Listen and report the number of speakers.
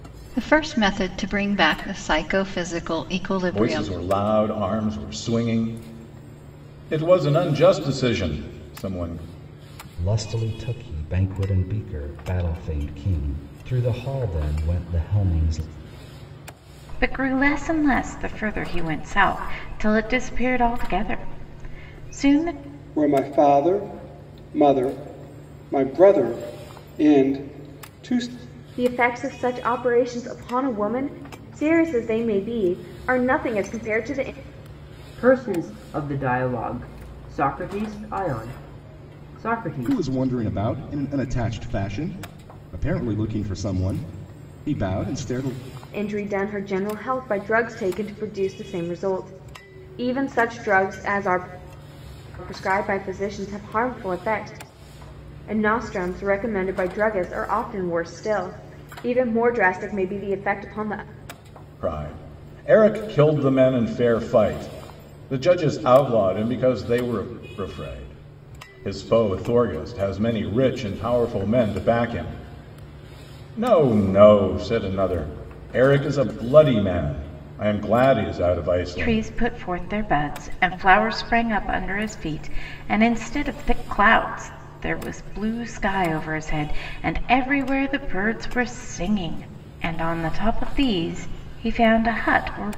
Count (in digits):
8